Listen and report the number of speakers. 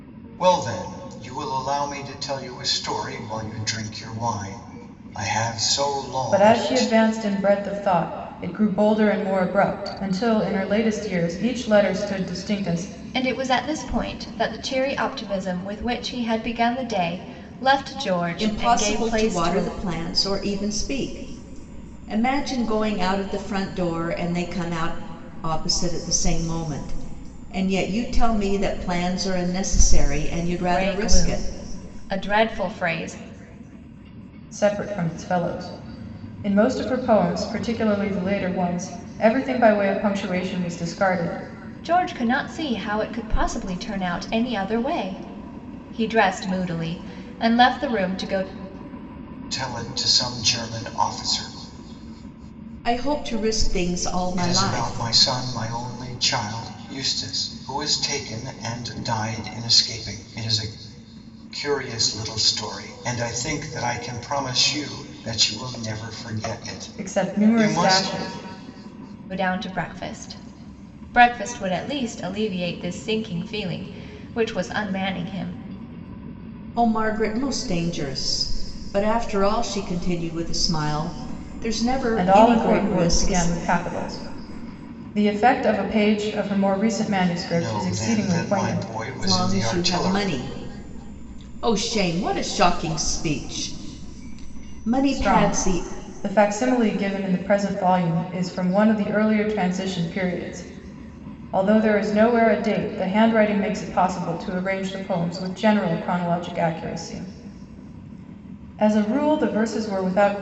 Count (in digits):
4